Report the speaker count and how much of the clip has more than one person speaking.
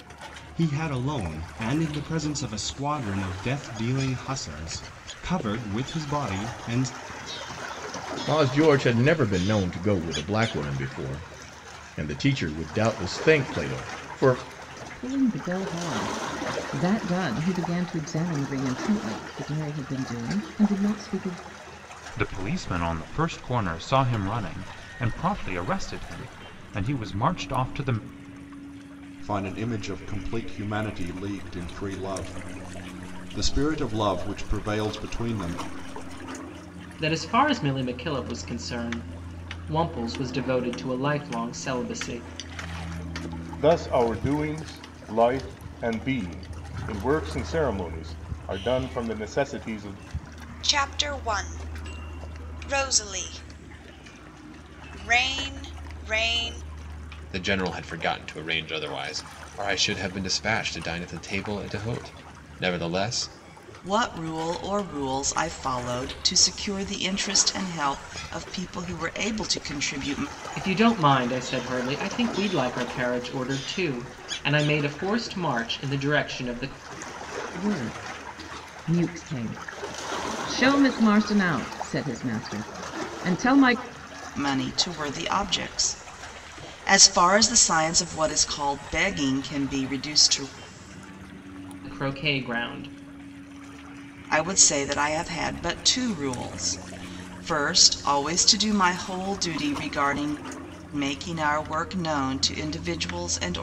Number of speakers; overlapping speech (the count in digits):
10, no overlap